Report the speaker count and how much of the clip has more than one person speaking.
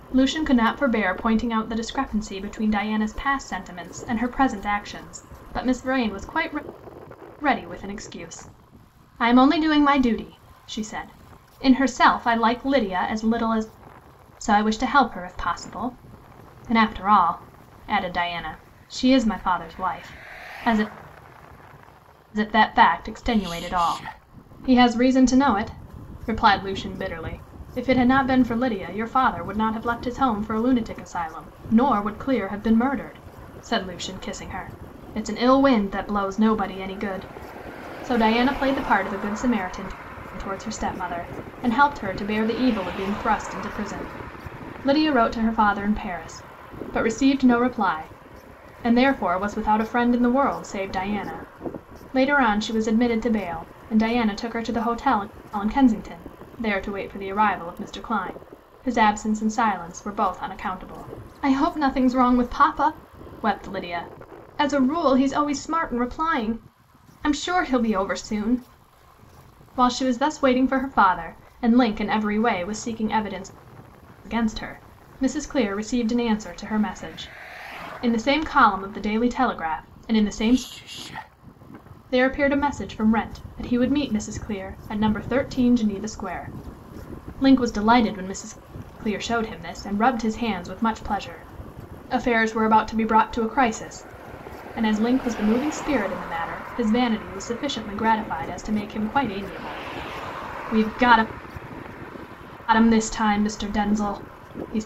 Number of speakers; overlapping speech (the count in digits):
1, no overlap